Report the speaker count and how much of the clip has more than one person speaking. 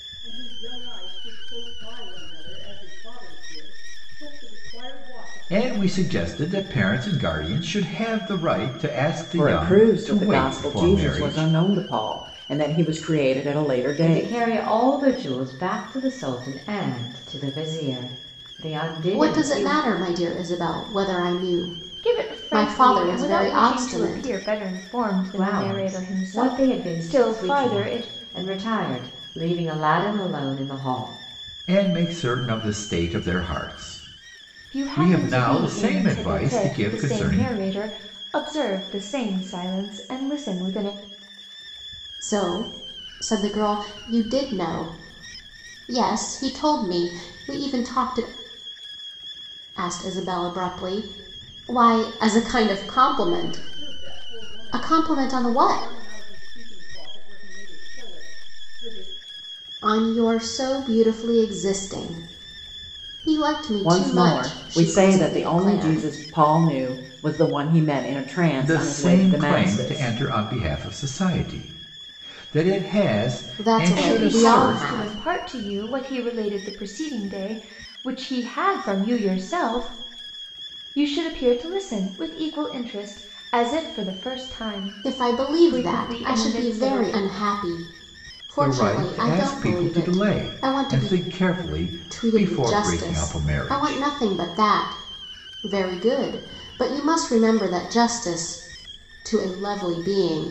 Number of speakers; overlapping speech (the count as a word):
six, about 27%